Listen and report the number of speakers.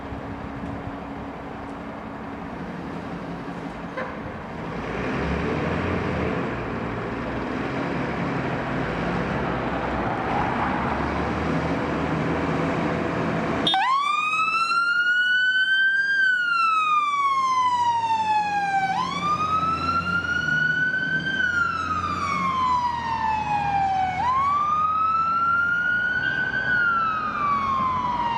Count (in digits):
0